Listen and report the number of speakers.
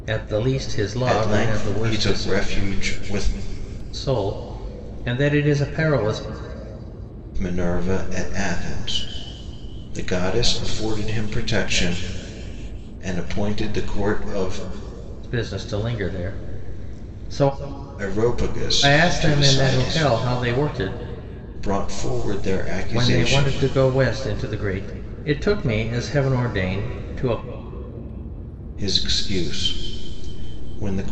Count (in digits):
2